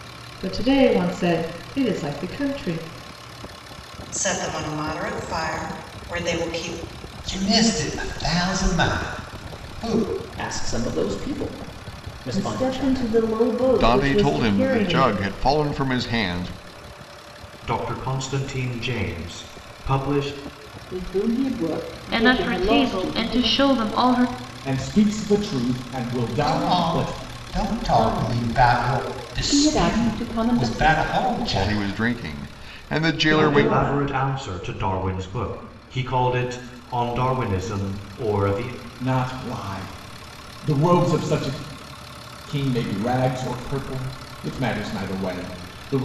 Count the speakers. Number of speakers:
10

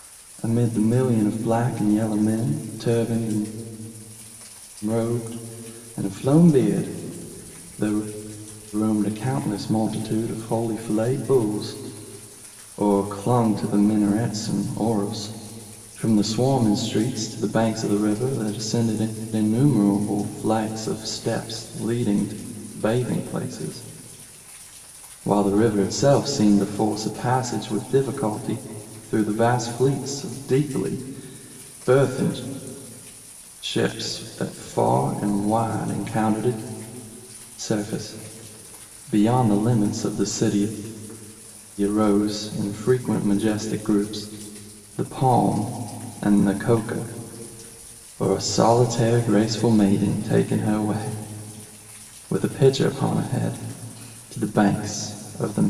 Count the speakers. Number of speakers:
1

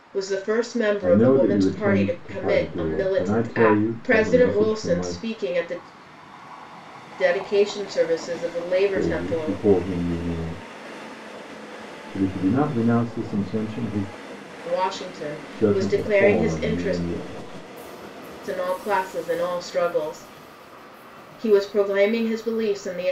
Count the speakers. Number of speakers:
2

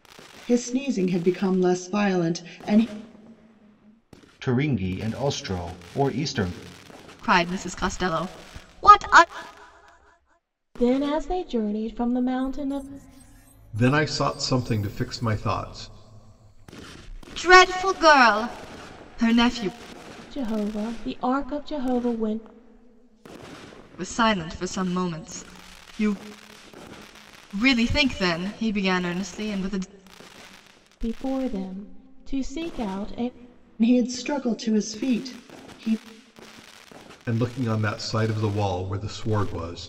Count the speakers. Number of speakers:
5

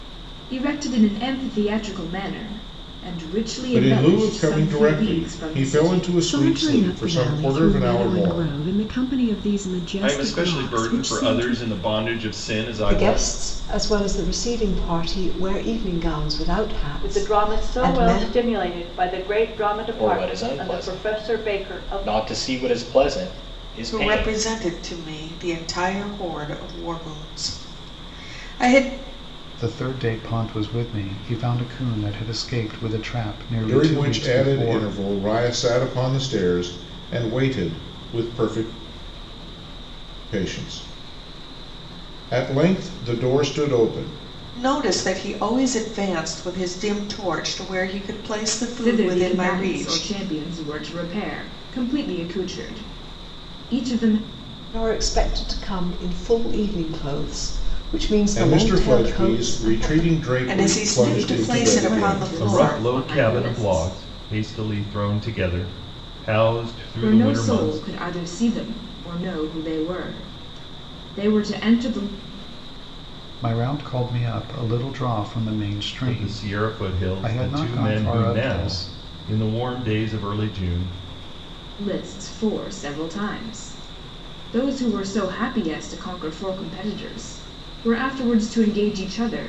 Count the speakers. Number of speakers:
9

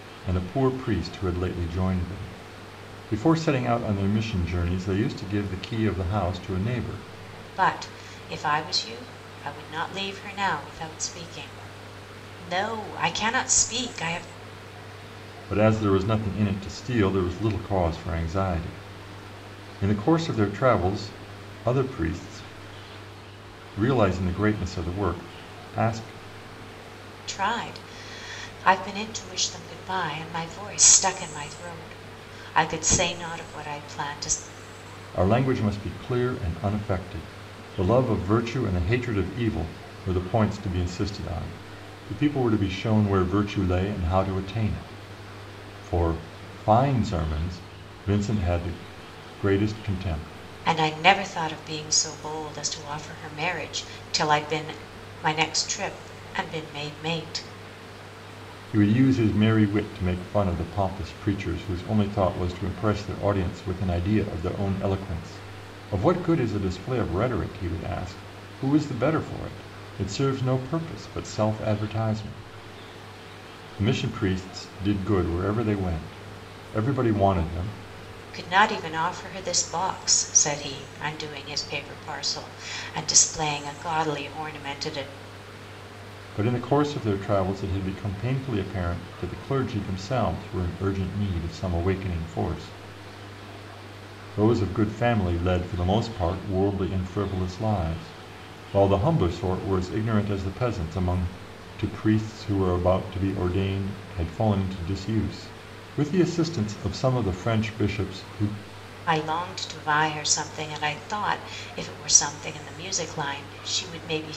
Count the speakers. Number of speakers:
2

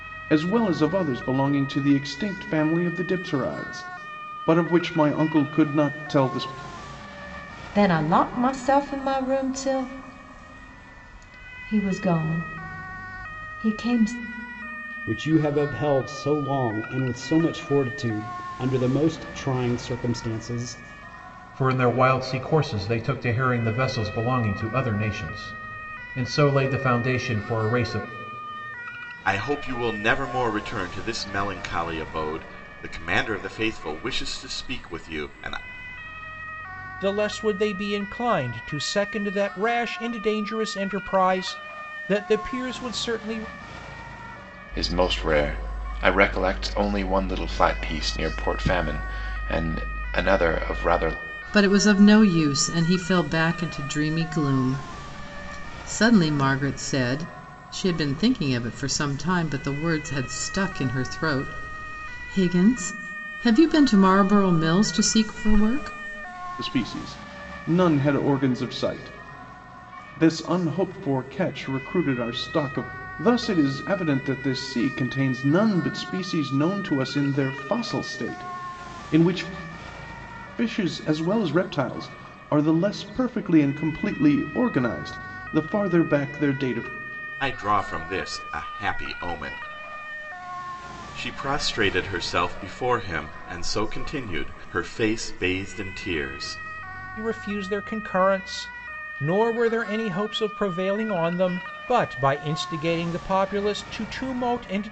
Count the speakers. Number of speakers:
8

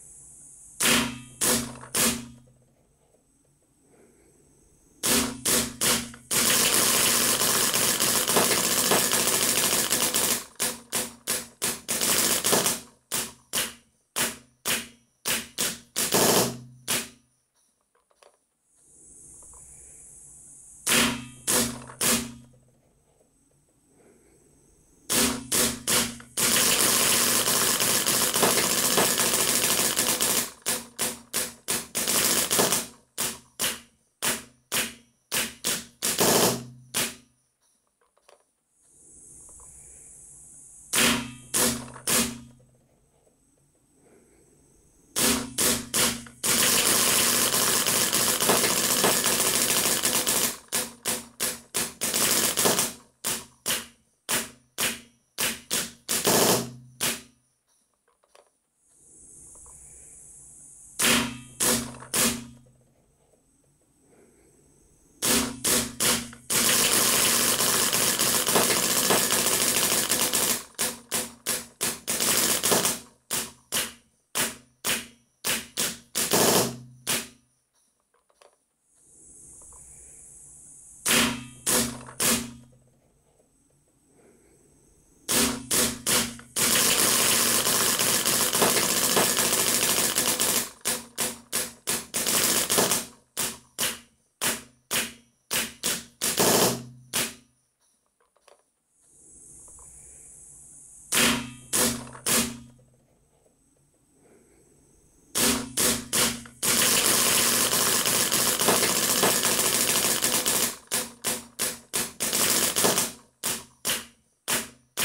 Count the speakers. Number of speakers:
0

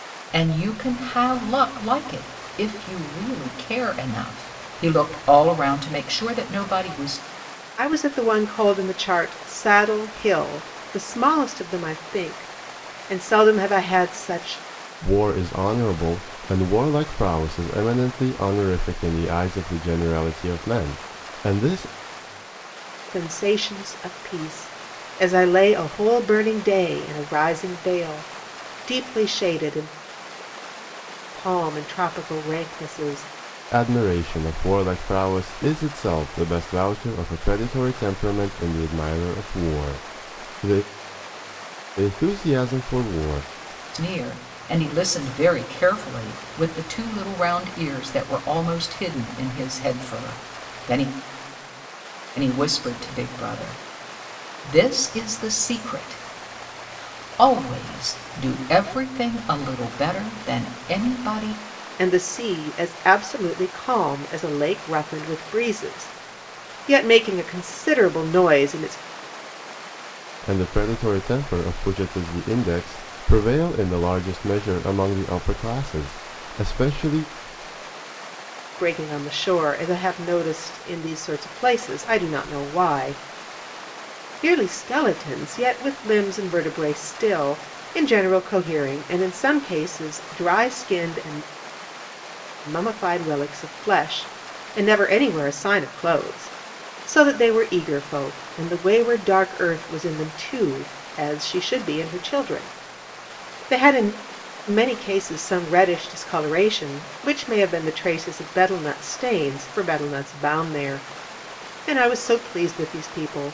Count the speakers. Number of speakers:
3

